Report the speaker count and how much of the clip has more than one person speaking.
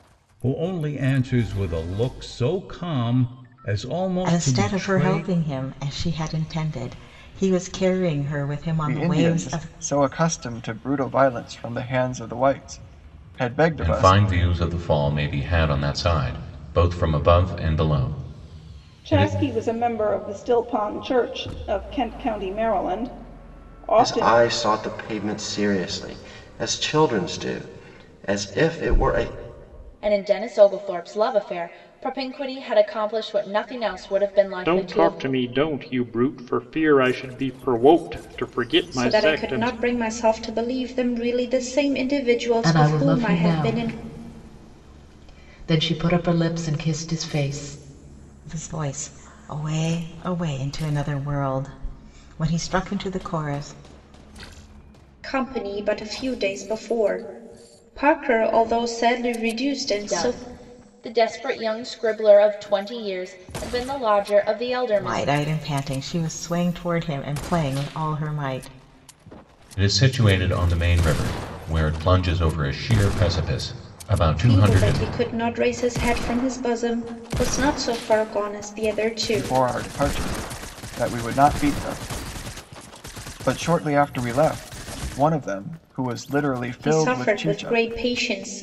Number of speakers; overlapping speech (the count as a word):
ten, about 10%